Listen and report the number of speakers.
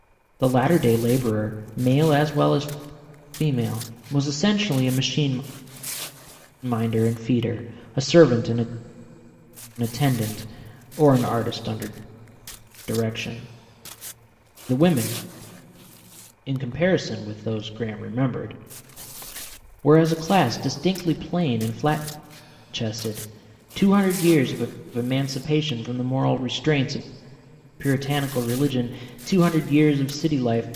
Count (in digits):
1